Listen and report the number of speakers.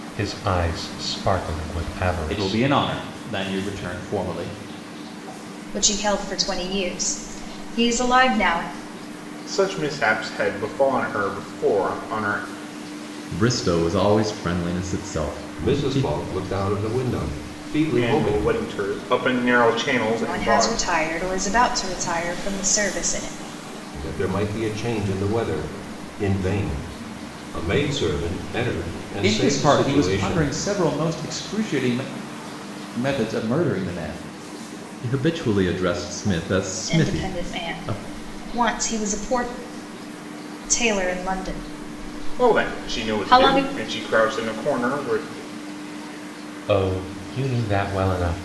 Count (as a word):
six